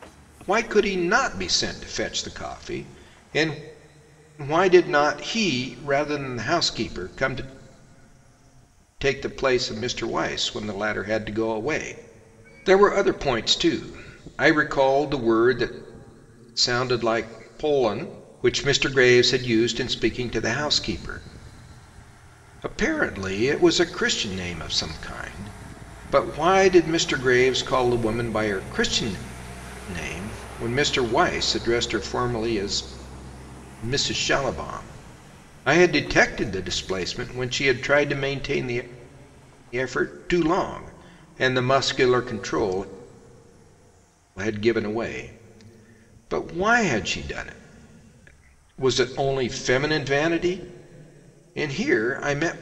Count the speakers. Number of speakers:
1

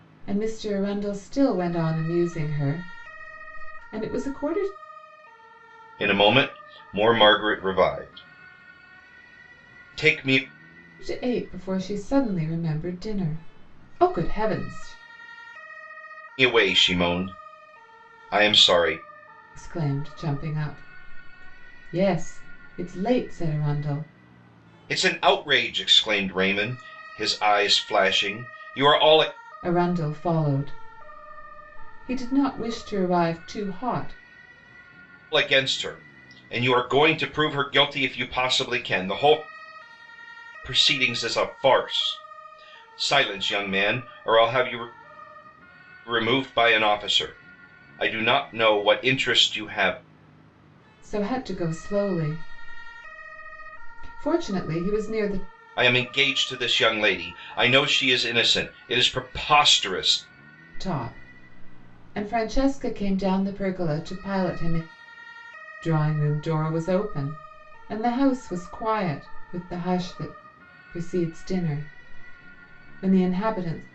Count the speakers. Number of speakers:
2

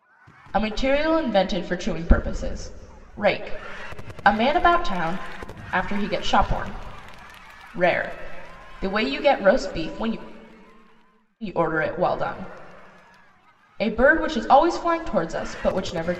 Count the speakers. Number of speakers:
1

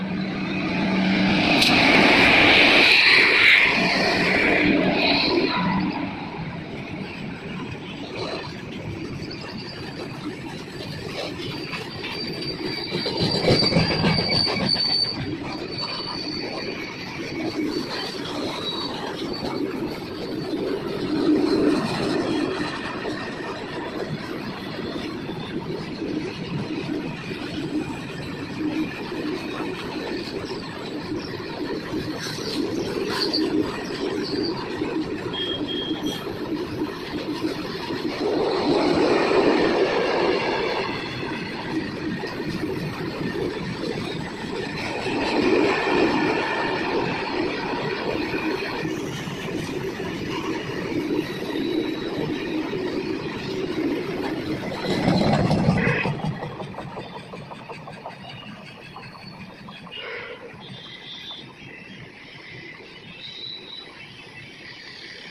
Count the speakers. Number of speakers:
0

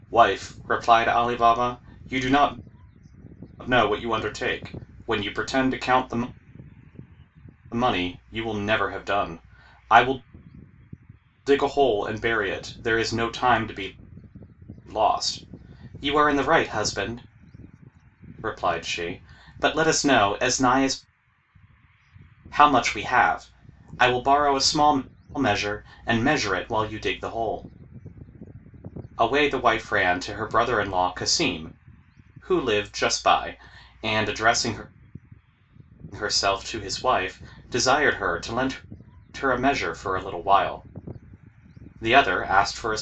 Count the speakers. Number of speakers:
1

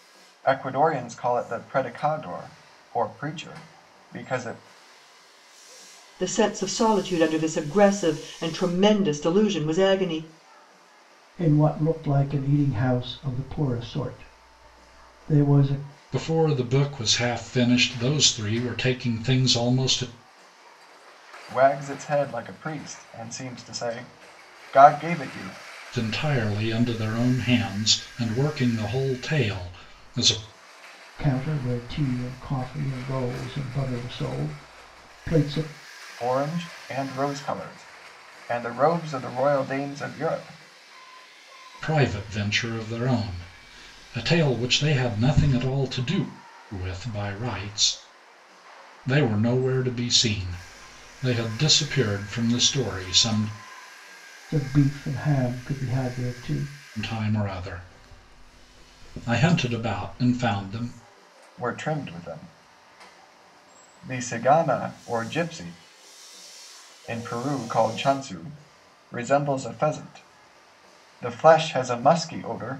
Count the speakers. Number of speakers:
4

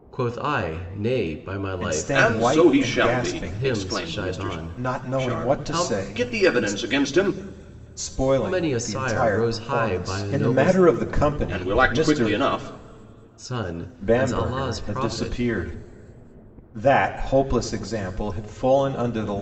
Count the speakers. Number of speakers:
3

